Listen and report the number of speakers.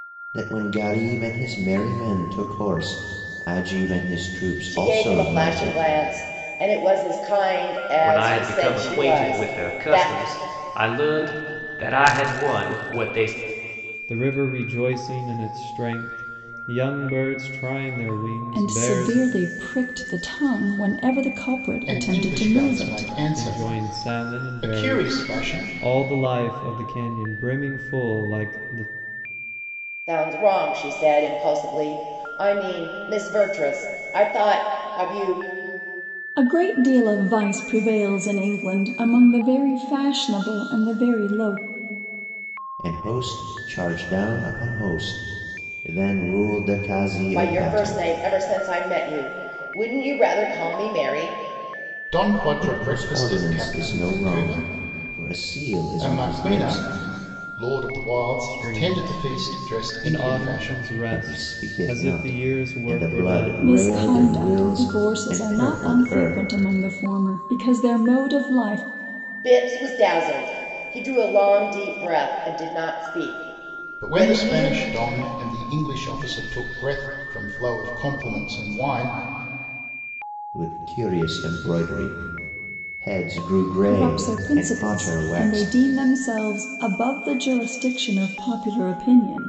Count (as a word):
six